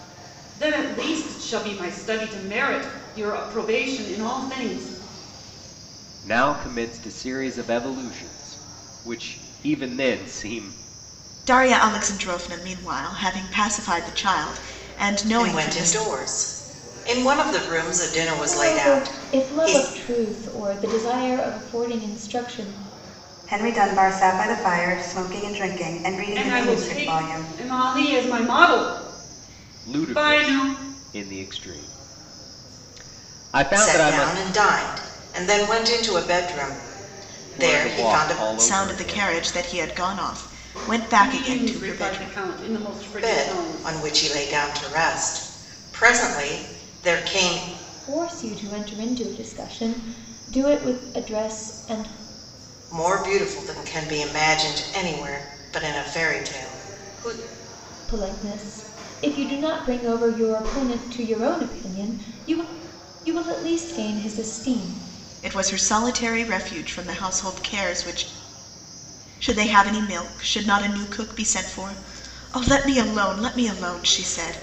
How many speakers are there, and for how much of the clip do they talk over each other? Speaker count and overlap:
six, about 11%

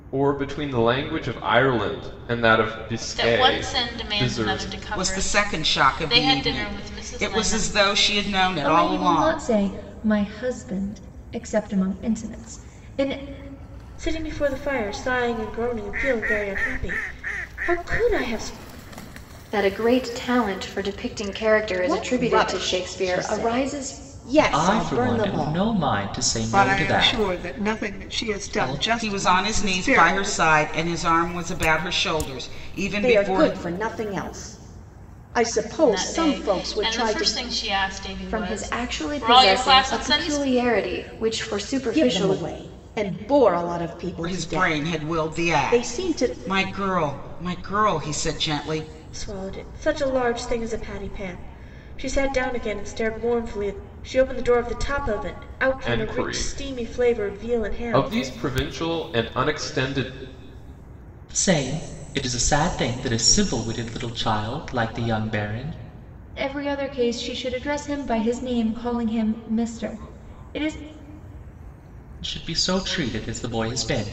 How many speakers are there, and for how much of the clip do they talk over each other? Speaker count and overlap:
nine, about 30%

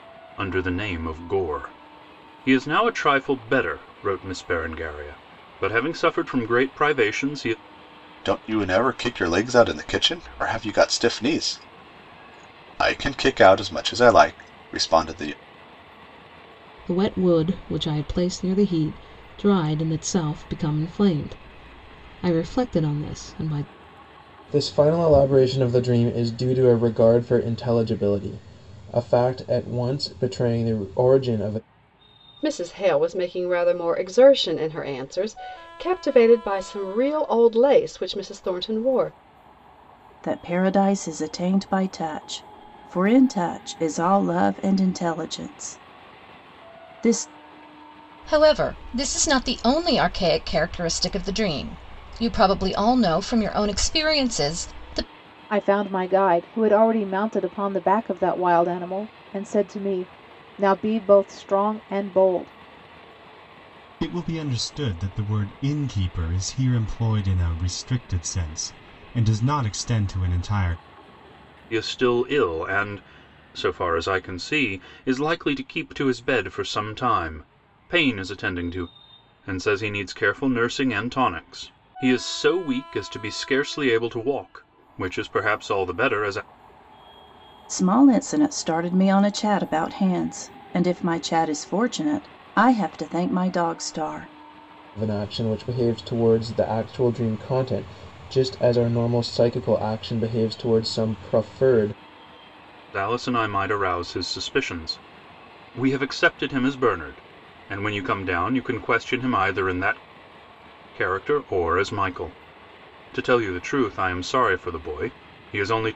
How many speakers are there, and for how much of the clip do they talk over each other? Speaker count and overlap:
nine, no overlap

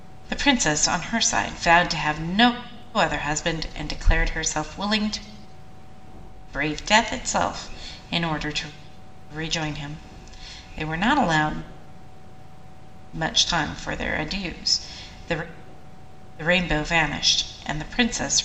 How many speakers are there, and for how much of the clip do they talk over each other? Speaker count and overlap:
one, no overlap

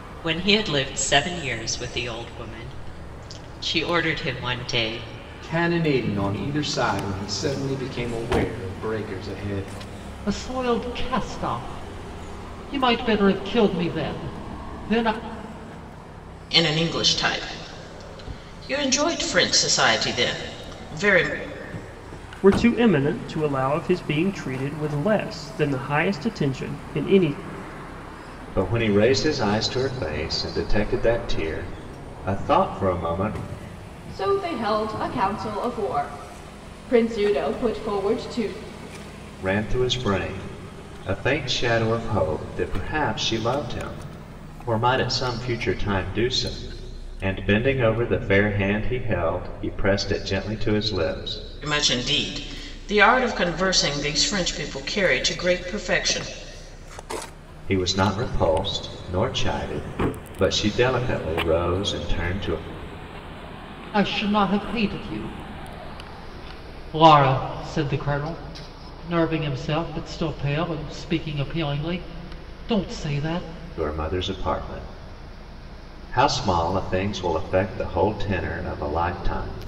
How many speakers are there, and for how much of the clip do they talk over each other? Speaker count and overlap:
seven, no overlap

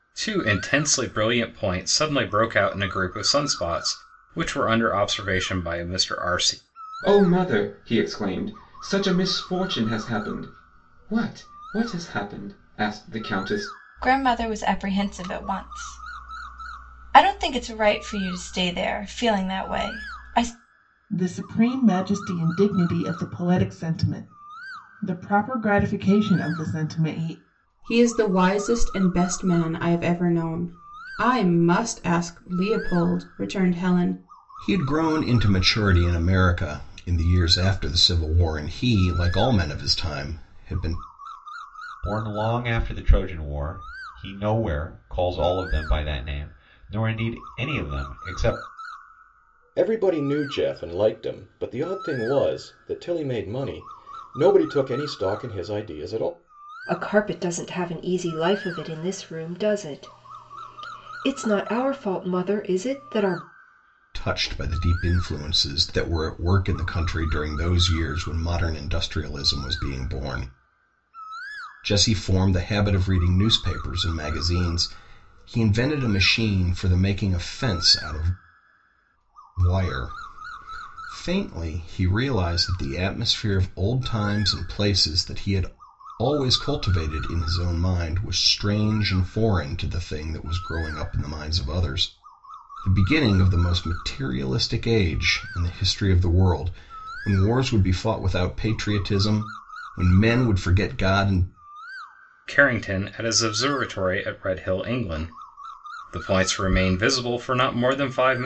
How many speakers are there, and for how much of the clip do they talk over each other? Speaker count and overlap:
nine, no overlap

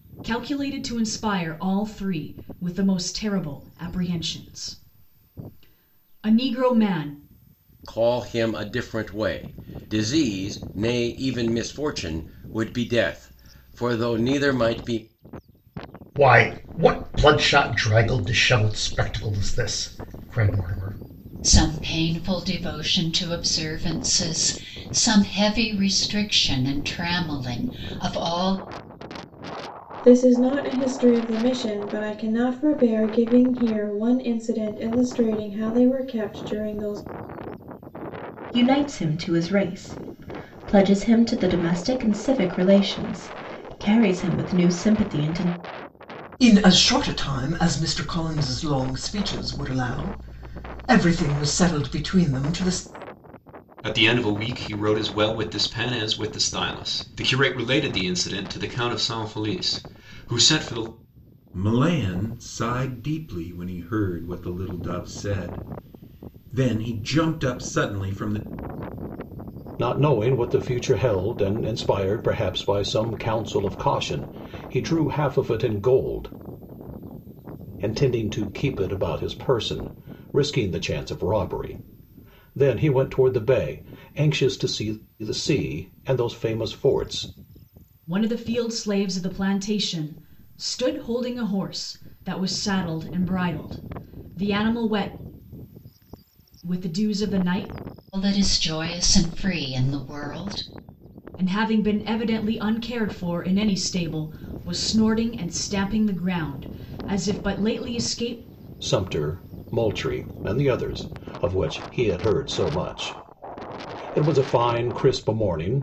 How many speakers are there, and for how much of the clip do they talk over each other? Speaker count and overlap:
ten, no overlap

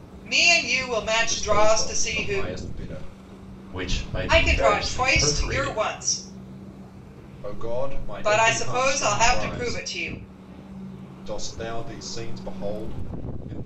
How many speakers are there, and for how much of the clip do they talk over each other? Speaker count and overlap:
three, about 33%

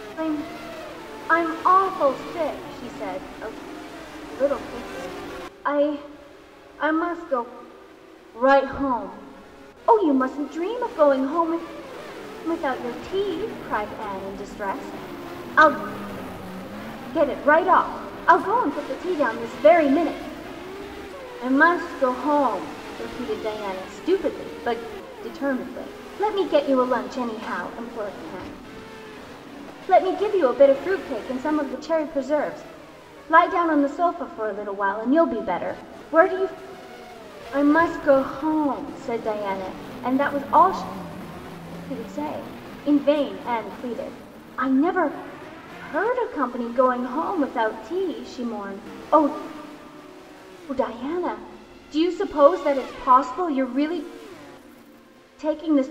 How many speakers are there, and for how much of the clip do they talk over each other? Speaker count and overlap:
one, no overlap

